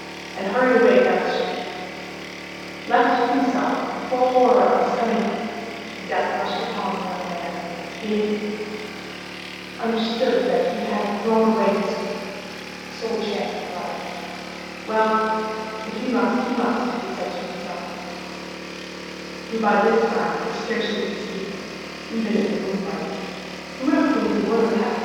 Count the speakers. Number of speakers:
1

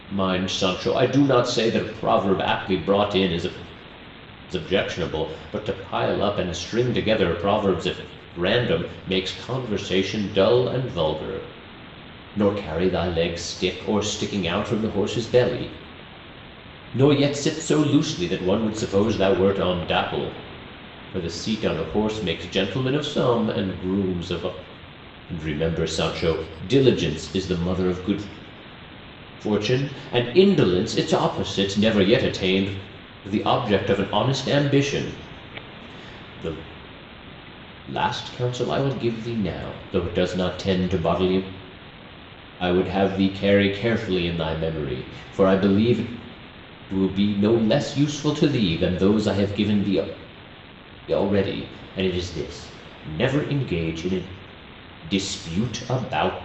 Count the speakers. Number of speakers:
1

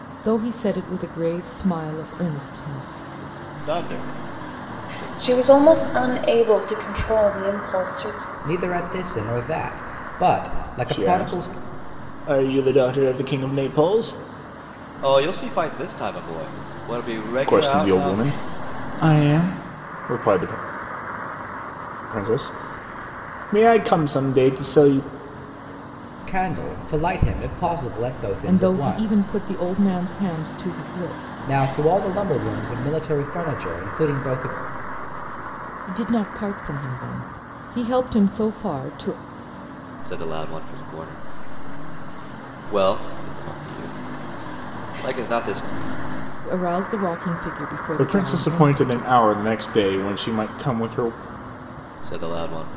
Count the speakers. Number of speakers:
5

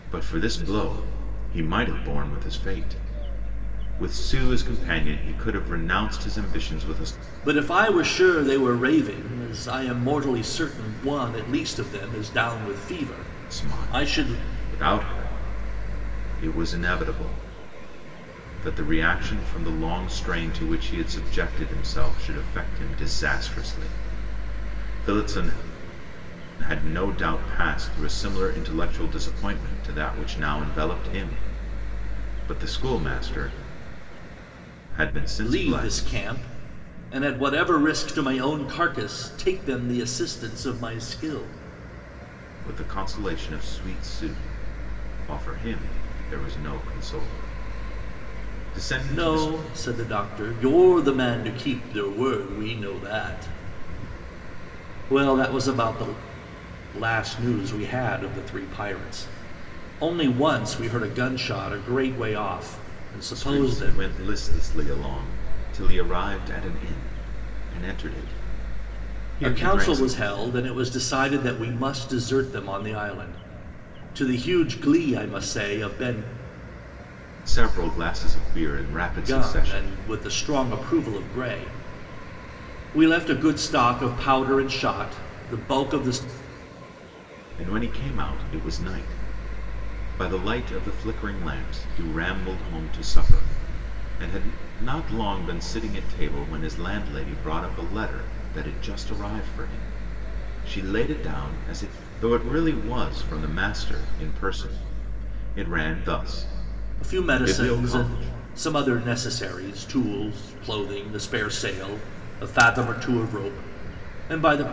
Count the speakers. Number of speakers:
2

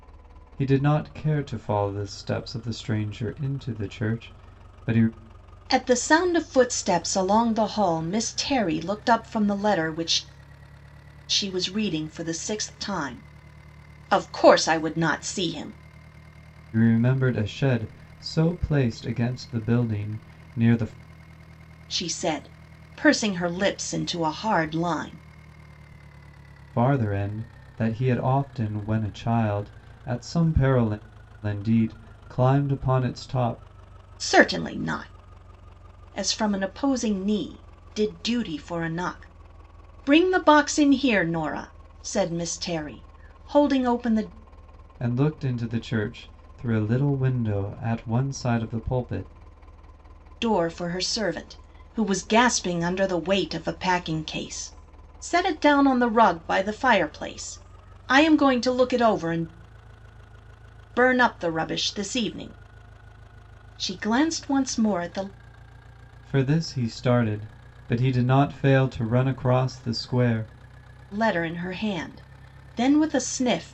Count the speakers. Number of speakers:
2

